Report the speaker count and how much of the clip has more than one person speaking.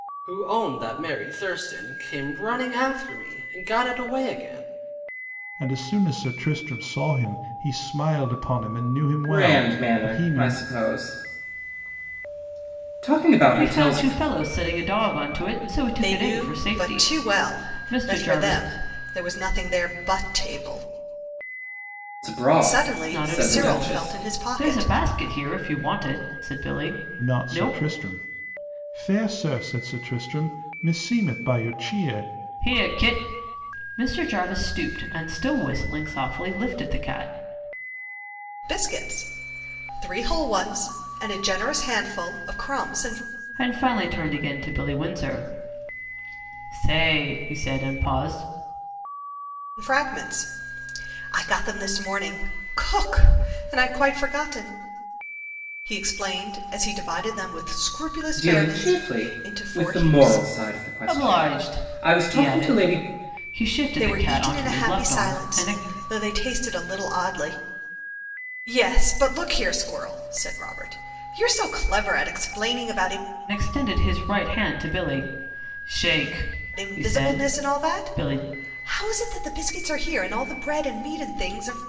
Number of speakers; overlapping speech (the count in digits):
5, about 19%